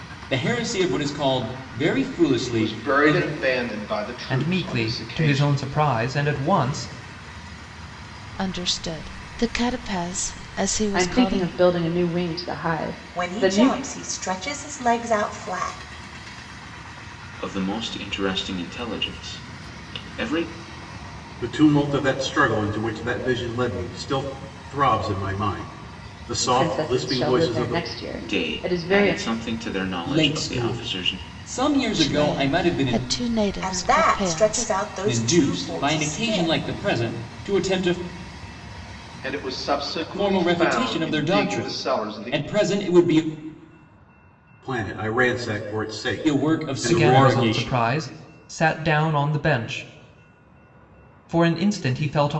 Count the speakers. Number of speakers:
8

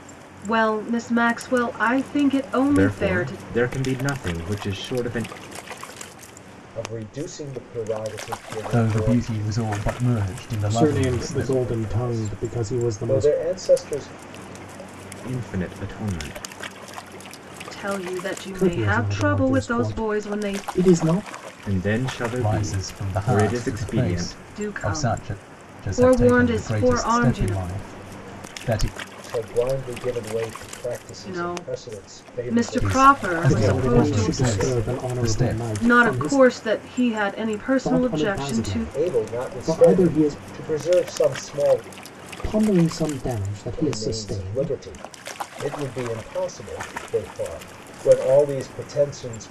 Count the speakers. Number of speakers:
5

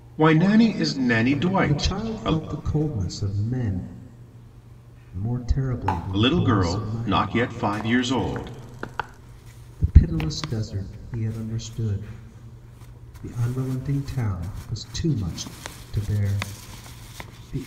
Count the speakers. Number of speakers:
2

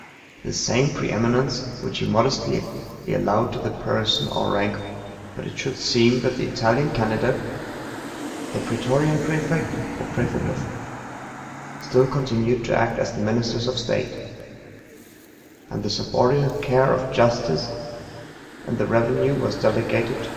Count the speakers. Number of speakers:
1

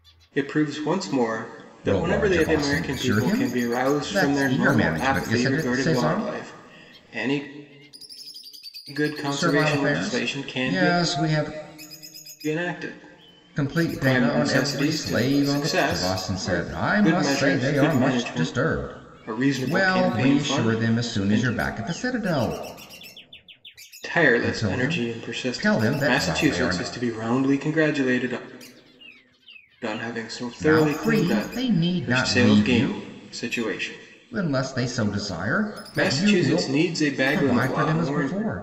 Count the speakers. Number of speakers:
2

